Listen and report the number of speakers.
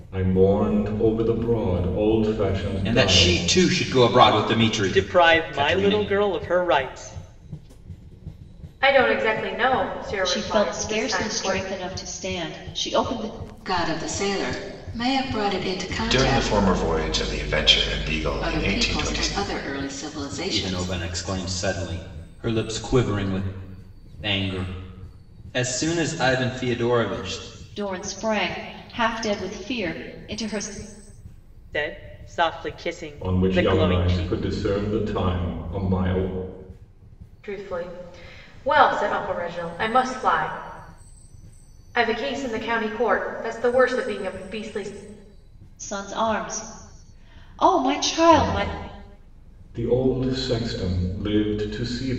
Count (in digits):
7